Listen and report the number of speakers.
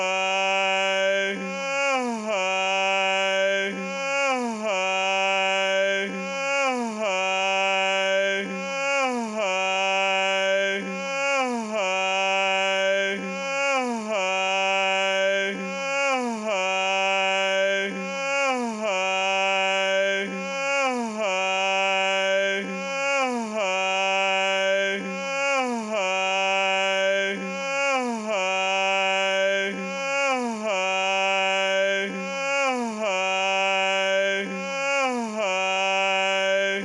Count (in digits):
0